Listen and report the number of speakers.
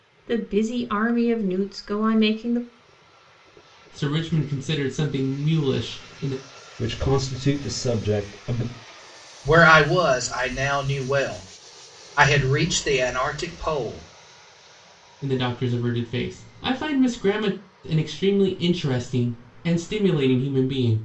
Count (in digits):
4